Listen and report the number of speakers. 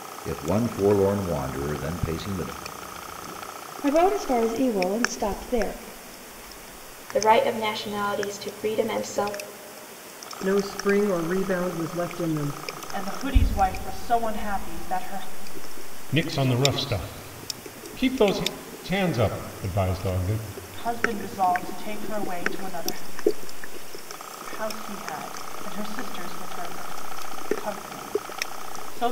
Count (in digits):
6